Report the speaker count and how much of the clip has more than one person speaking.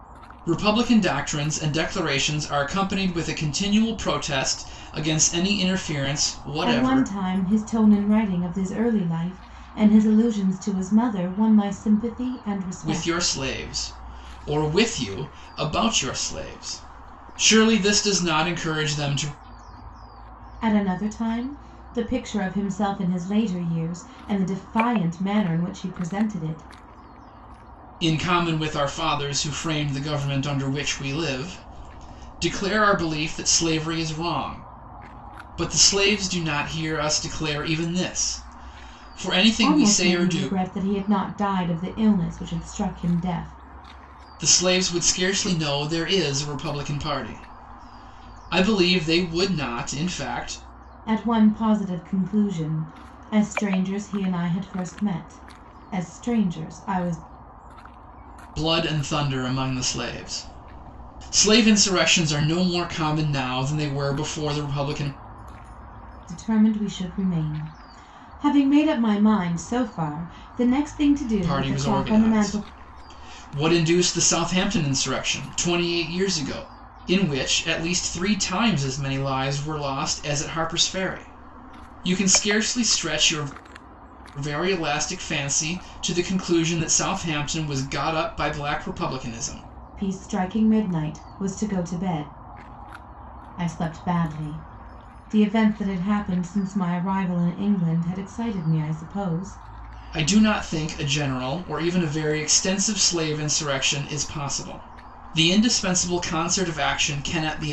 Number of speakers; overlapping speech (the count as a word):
two, about 3%